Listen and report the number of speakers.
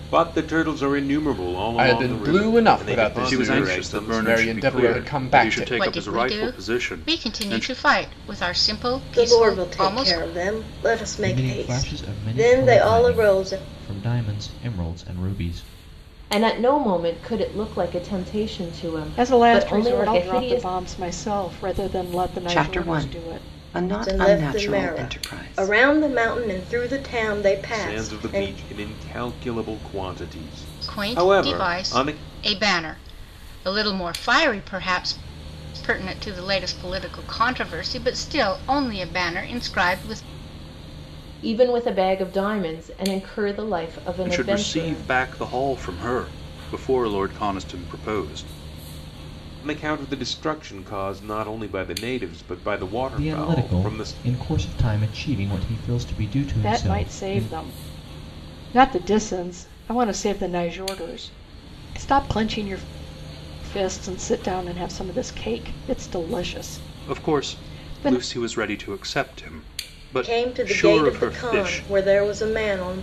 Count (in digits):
9